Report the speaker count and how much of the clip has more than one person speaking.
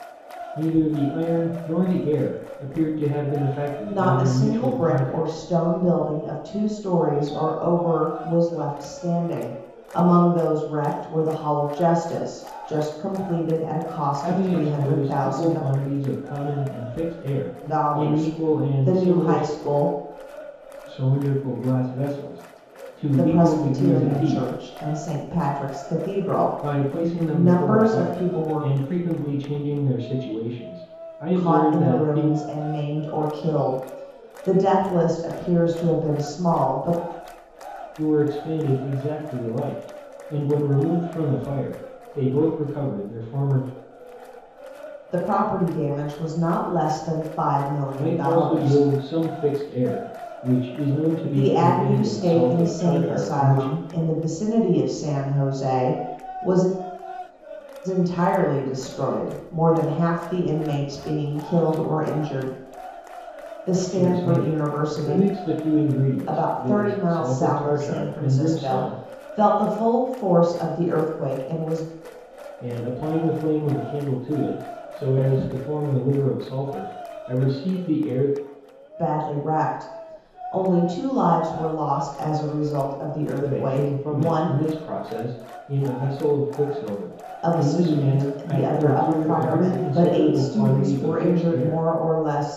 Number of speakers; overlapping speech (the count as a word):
two, about 24%